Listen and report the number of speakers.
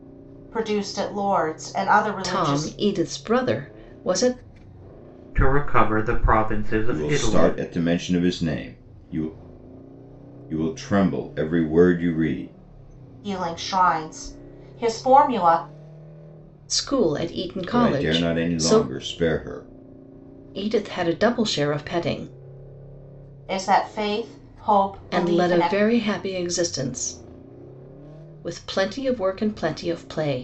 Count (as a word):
four